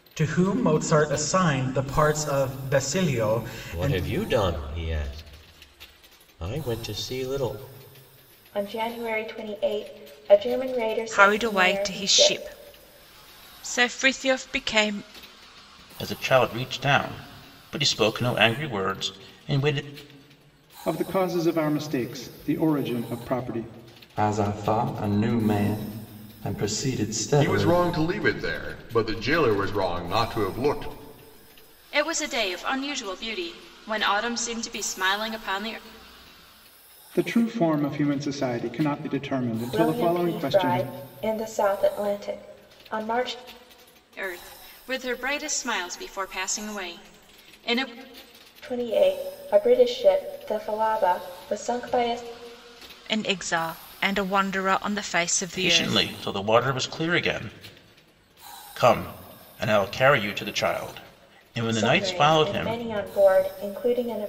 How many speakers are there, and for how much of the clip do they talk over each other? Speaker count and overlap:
nine, about 8%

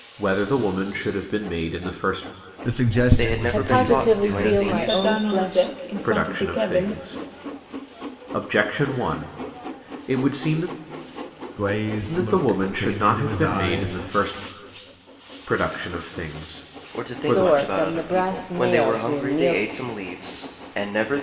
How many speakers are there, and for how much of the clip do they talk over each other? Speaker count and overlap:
five, about 39%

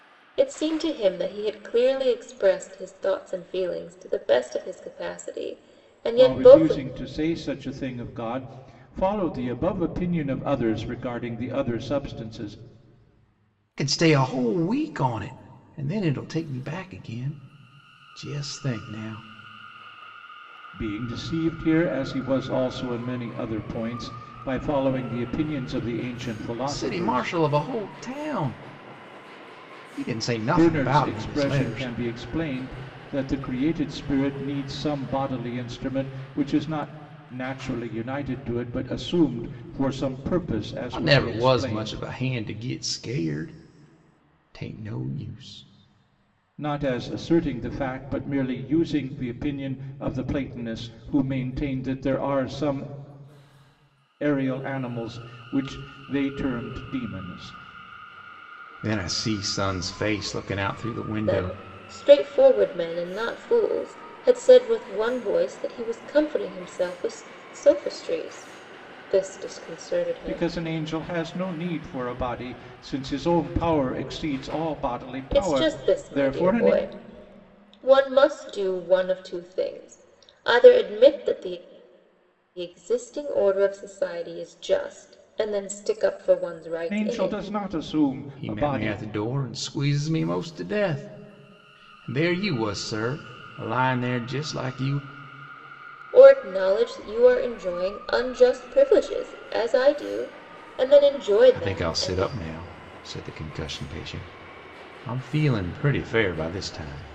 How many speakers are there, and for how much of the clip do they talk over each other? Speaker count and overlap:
three, about 8%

